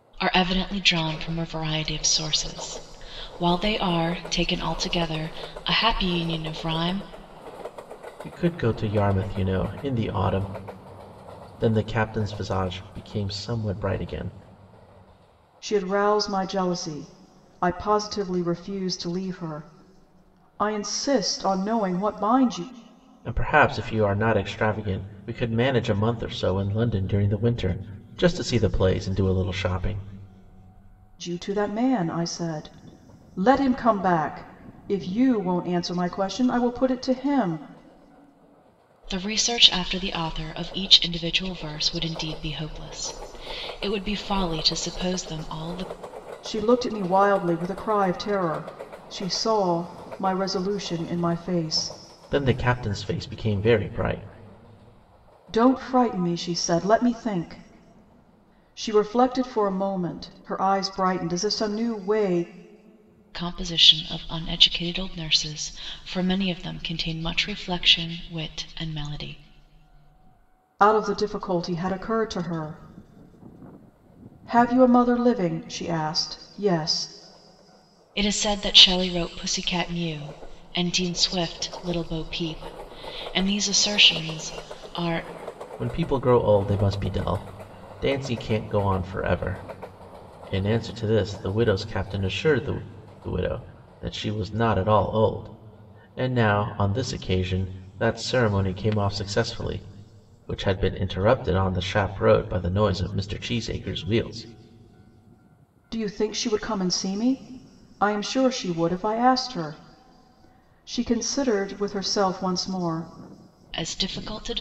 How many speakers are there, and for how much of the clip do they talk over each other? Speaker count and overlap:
three, no overlap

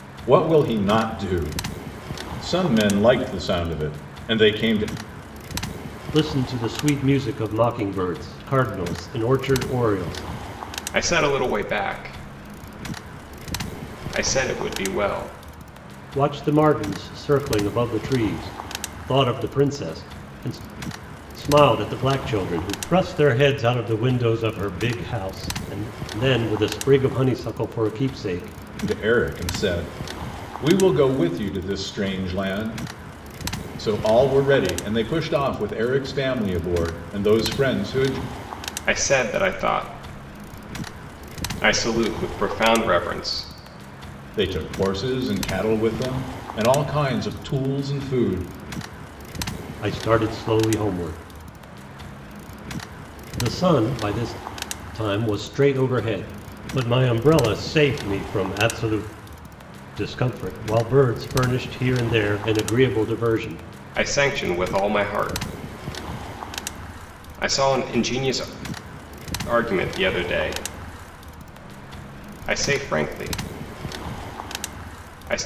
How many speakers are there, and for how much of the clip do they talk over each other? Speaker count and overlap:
three, no overlap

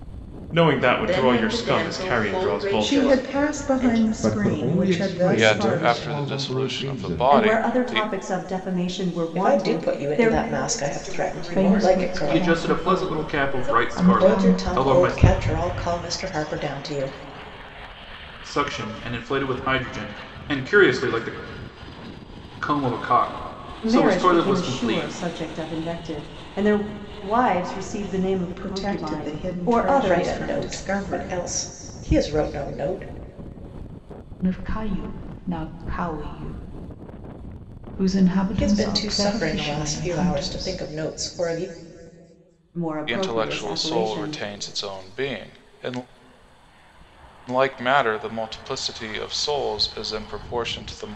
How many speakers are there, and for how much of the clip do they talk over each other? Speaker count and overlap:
ten, about 40%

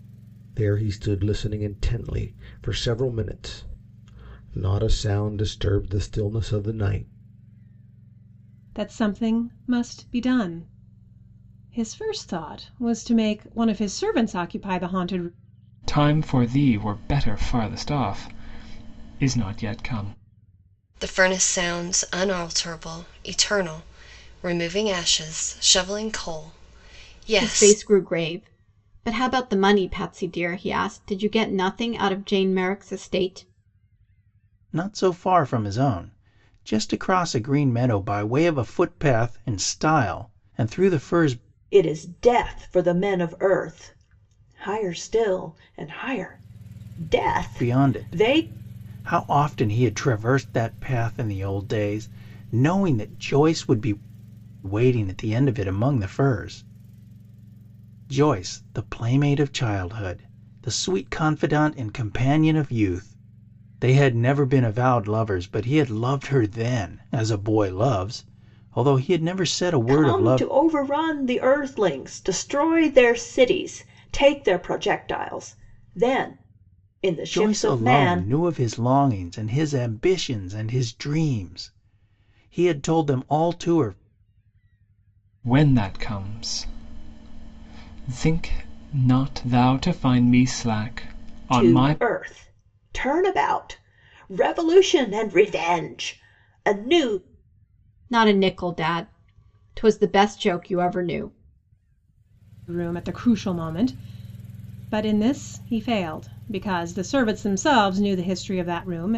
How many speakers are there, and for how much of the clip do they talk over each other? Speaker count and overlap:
seven, about 3%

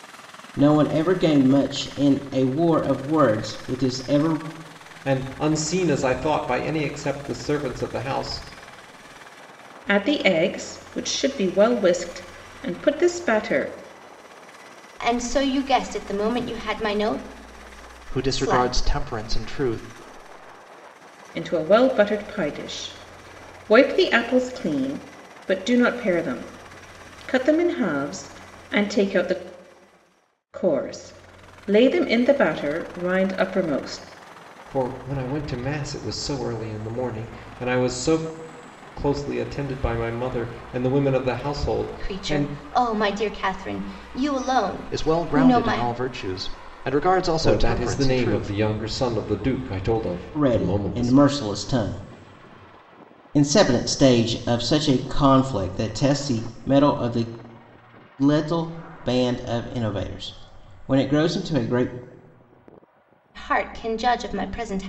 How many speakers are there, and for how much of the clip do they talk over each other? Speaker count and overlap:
five, about 7%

